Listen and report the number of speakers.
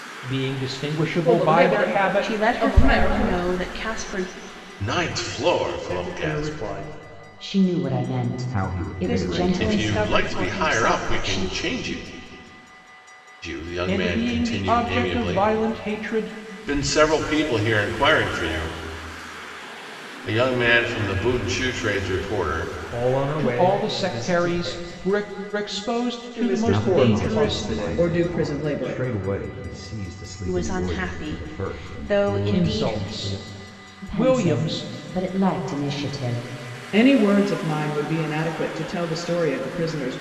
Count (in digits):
7